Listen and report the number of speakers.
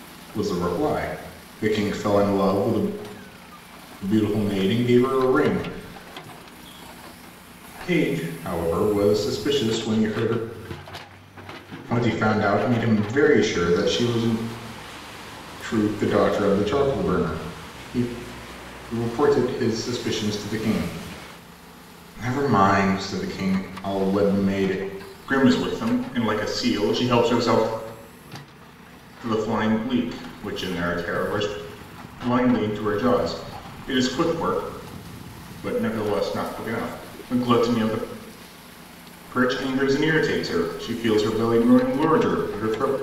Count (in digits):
1